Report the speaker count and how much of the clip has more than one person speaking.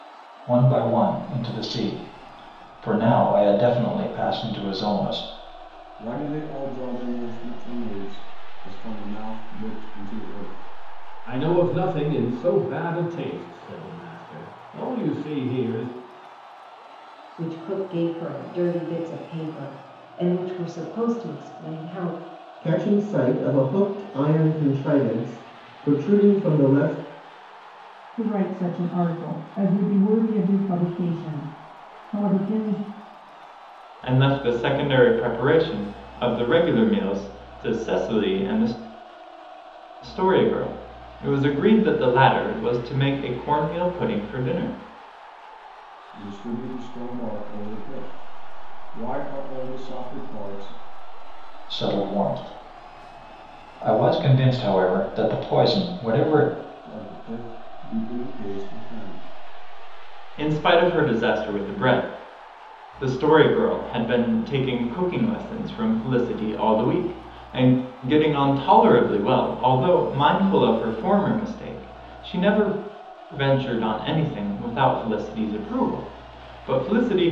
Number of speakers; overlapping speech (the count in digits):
7, no overlap